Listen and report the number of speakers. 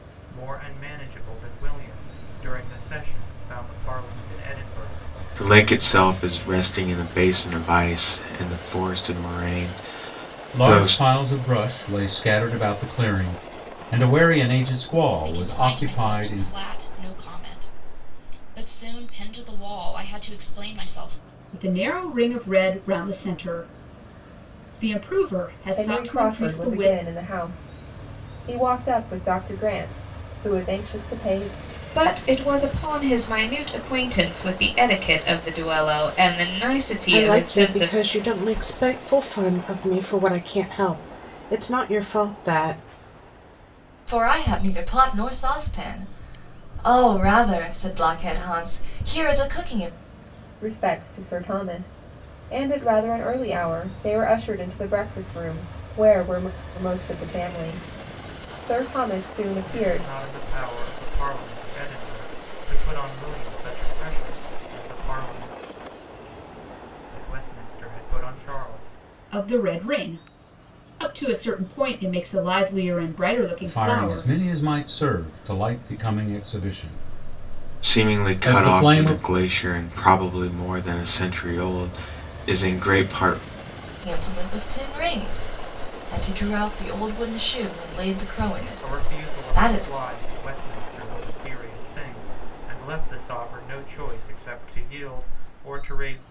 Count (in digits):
9